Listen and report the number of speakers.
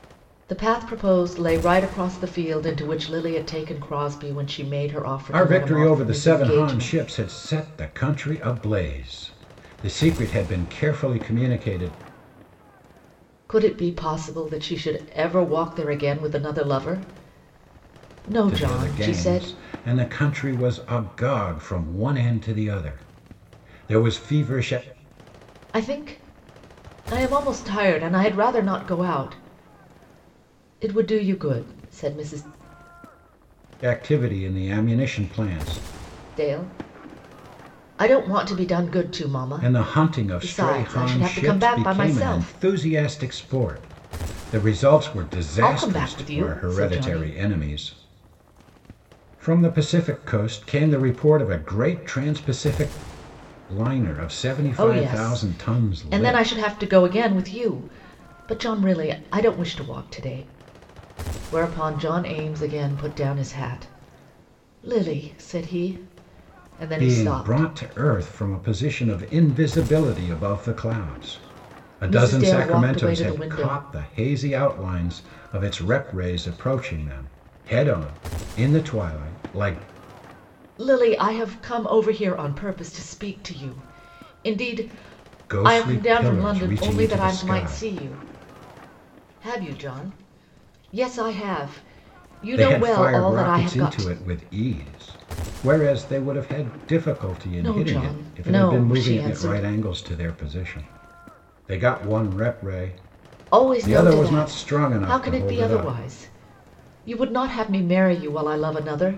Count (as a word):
two